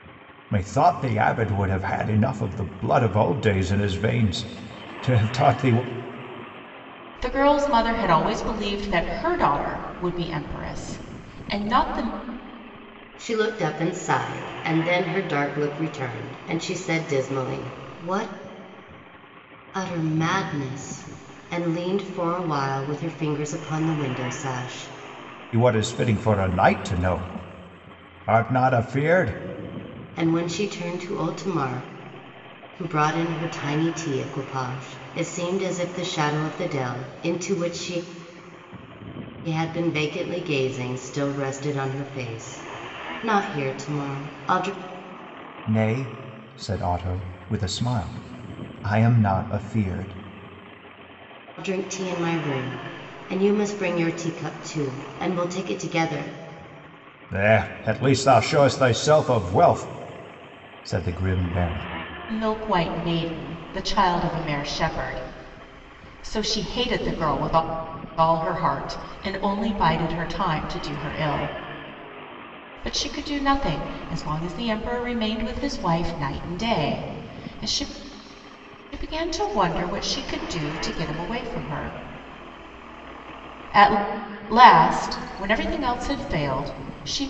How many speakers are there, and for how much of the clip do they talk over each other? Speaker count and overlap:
3, no overlap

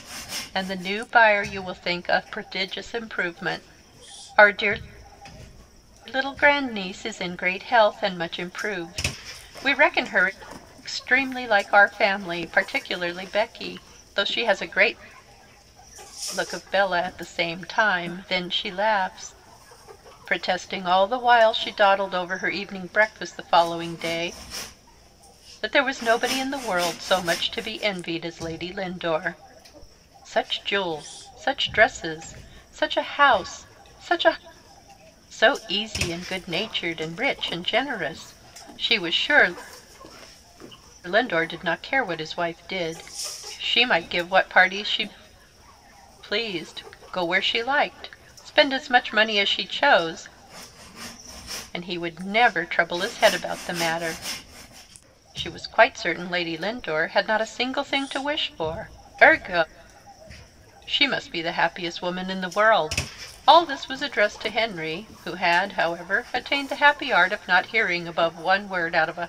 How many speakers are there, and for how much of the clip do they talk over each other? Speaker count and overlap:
1, no overlap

